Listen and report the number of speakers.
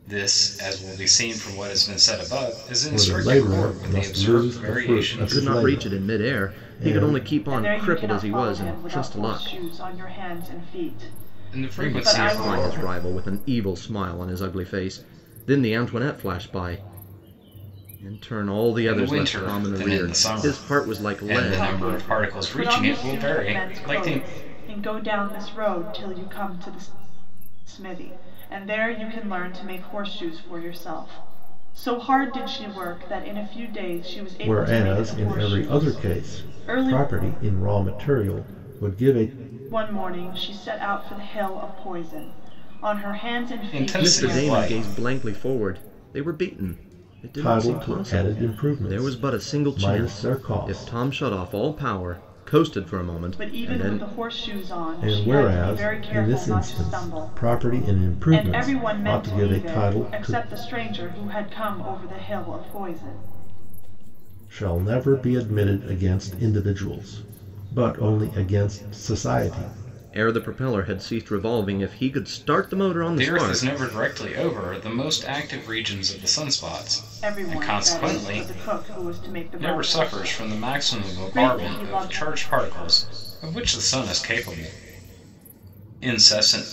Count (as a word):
four